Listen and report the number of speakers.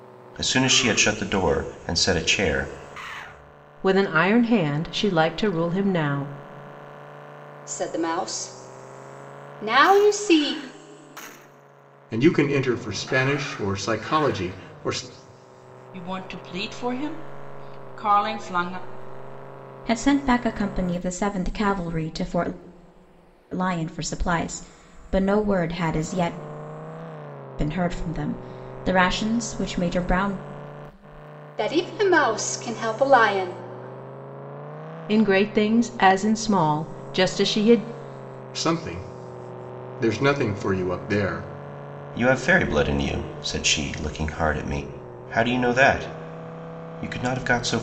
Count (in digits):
6